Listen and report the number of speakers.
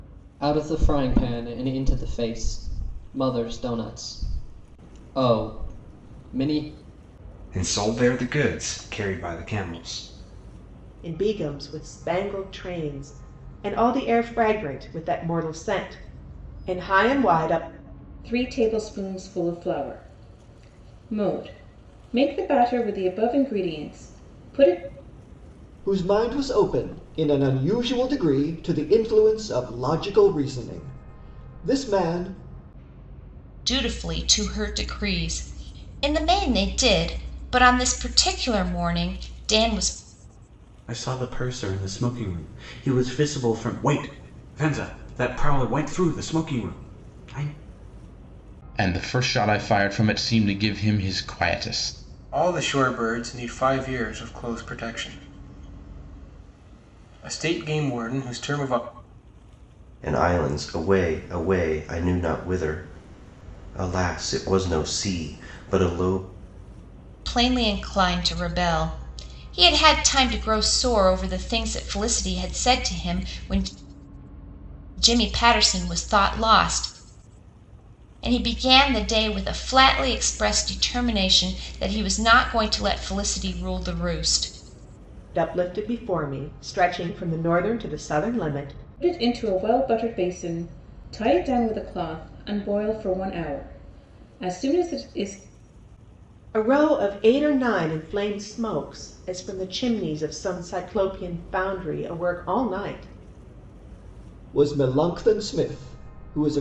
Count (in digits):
10